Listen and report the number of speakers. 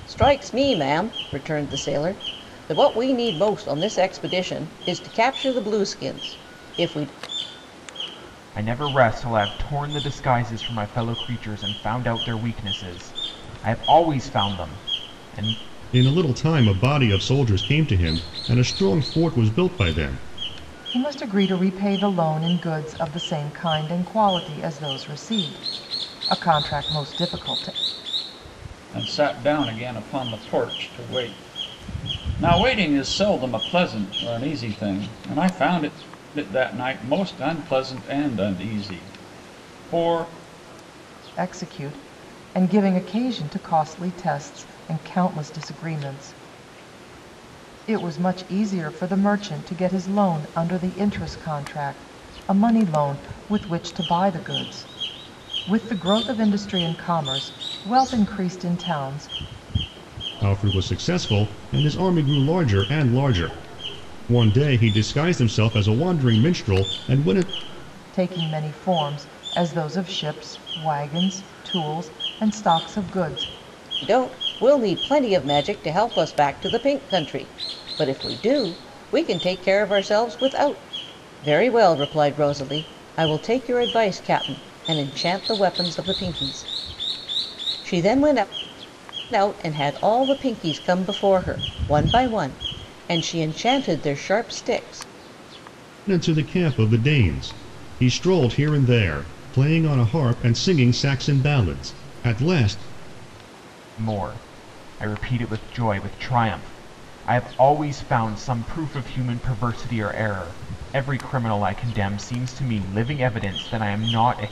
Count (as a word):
five